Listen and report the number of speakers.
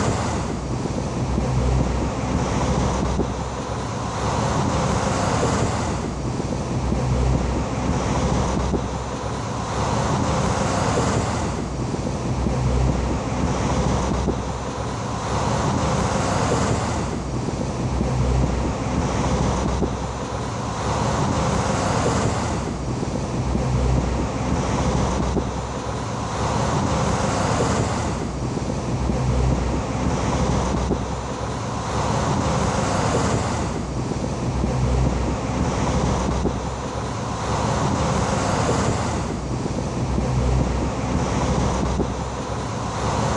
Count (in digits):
0